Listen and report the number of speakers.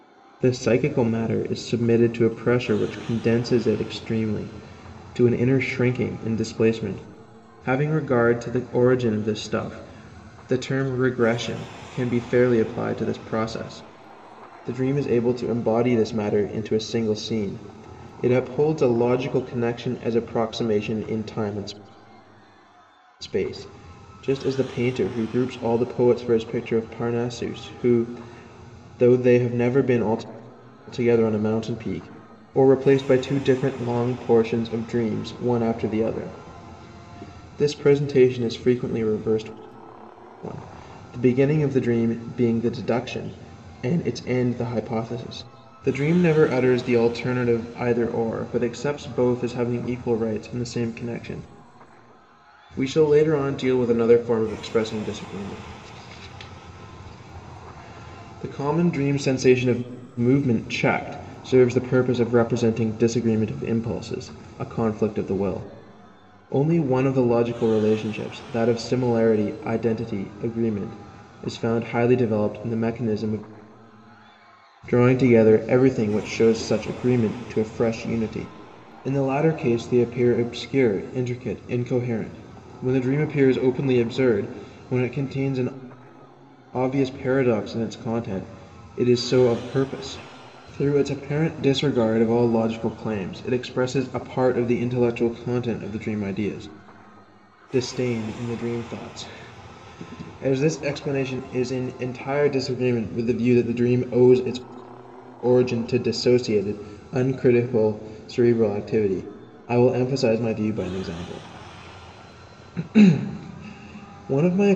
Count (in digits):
1